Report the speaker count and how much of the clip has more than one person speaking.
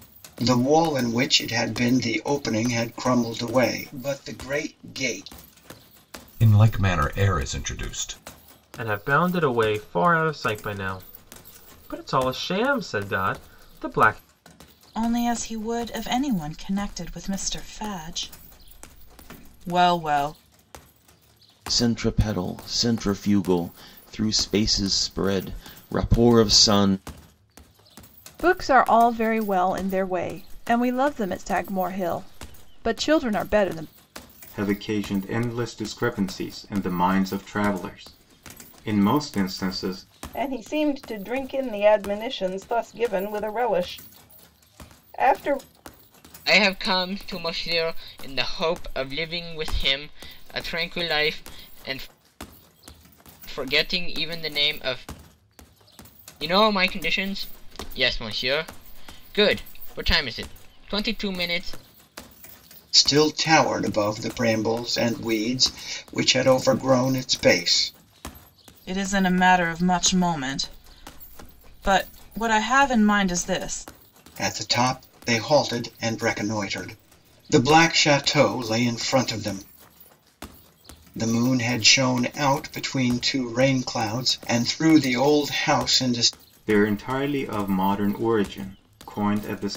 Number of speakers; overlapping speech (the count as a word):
nine, no overlap